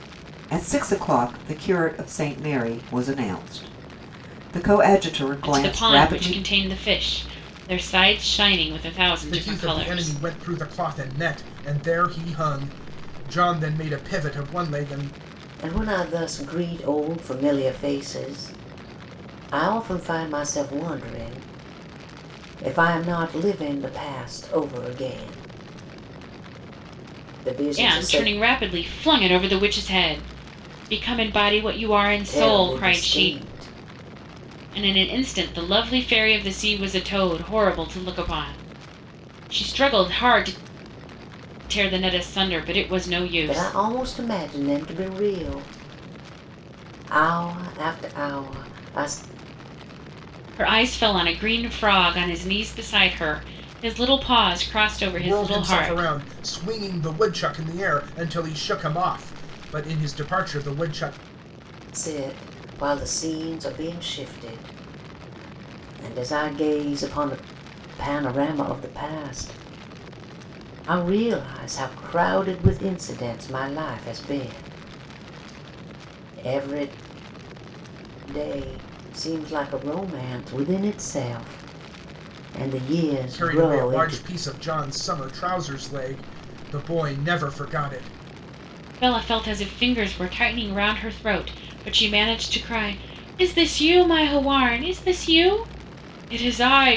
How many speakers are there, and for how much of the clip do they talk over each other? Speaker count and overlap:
four, about 6%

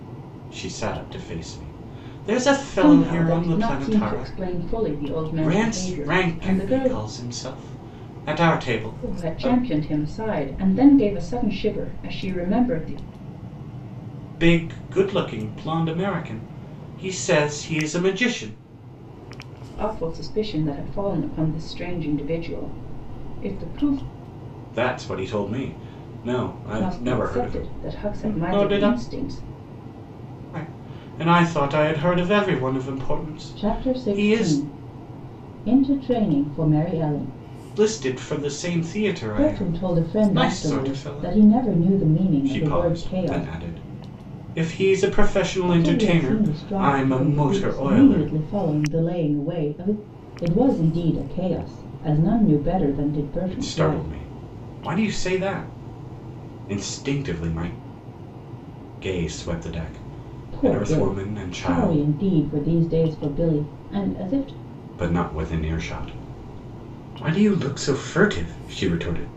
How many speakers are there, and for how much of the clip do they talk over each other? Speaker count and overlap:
two, about 22%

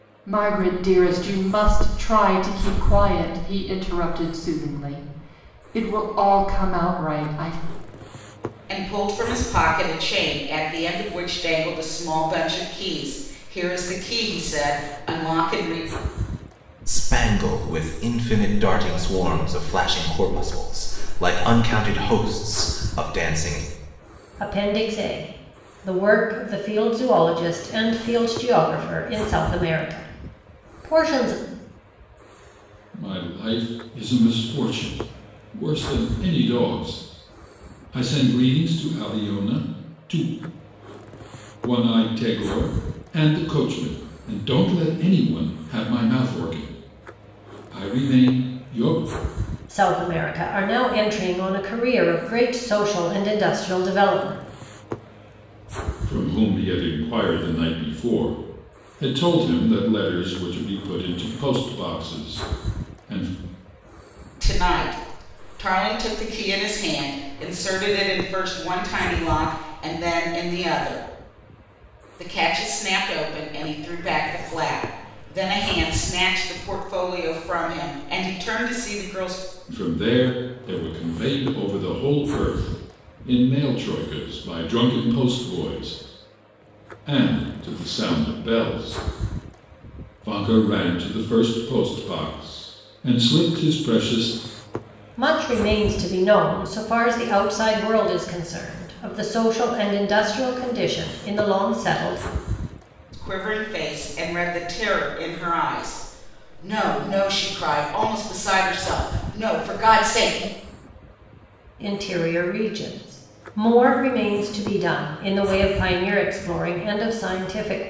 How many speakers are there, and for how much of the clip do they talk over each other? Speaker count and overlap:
five, no overlap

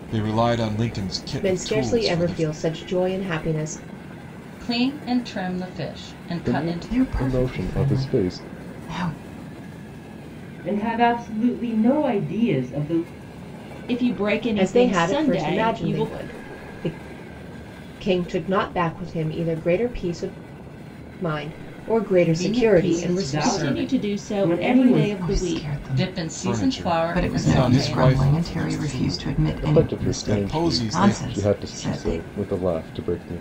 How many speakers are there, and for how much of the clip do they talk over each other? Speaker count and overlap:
seven, about 44%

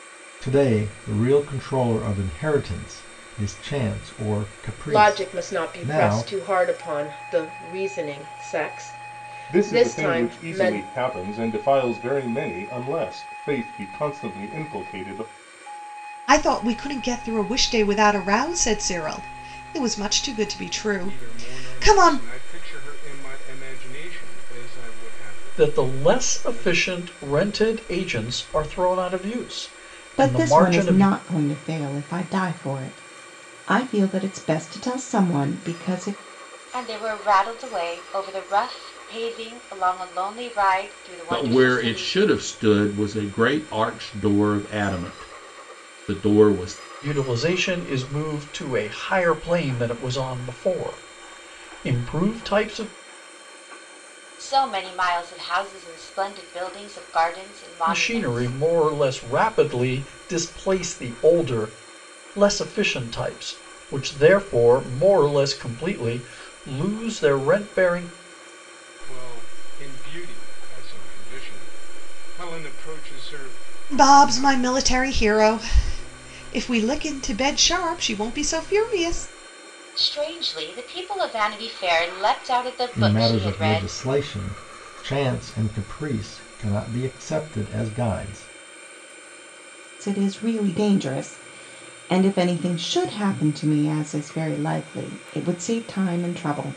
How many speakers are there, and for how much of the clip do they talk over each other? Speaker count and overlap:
nine, about 10%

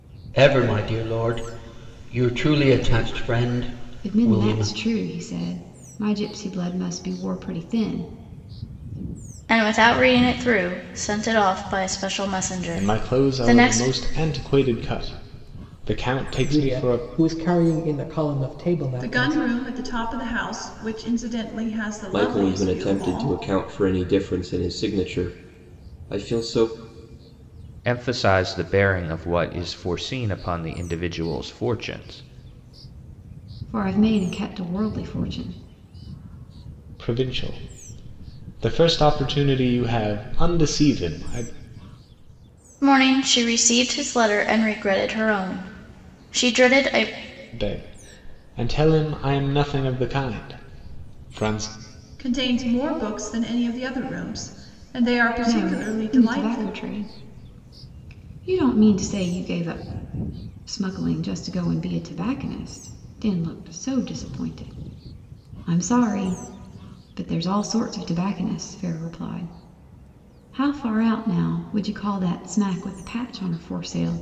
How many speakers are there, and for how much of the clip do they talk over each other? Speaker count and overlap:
eight, about 8%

